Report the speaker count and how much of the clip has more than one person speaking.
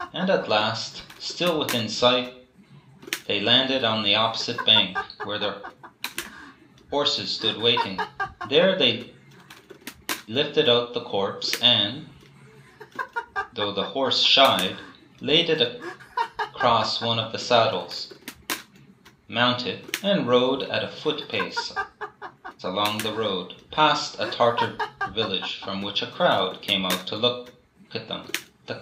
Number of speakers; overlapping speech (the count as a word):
one, no overlap